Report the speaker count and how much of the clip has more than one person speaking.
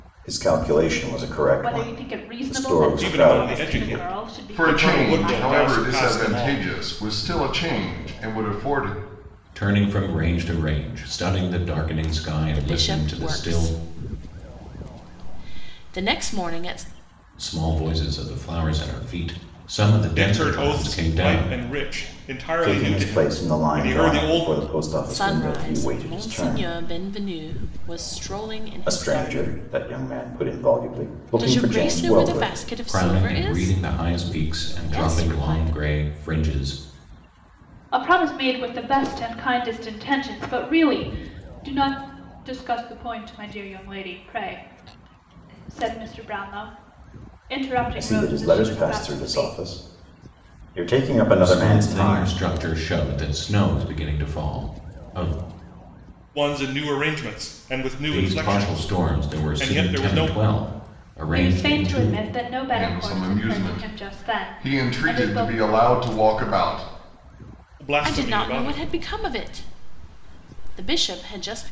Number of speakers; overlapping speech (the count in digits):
6, about 37%